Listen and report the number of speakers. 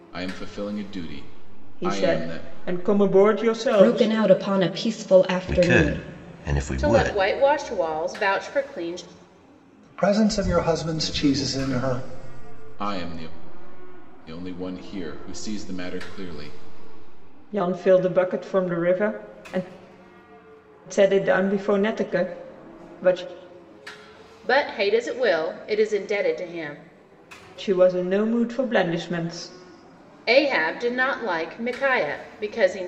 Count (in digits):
6